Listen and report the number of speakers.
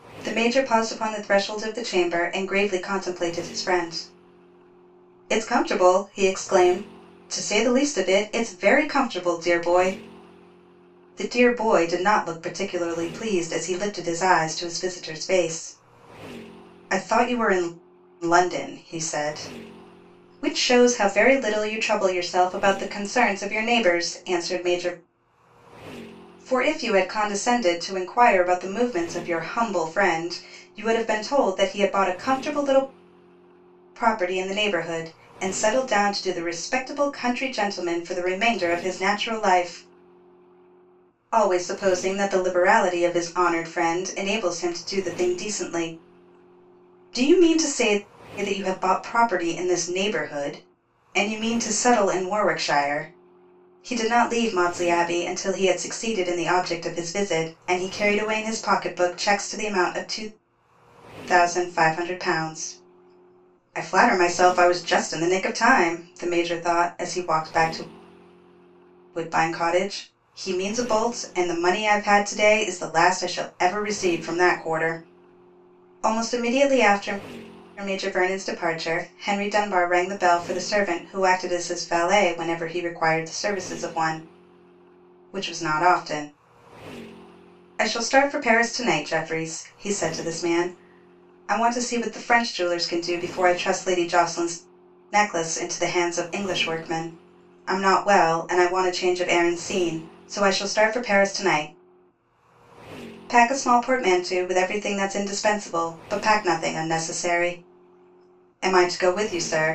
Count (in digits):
1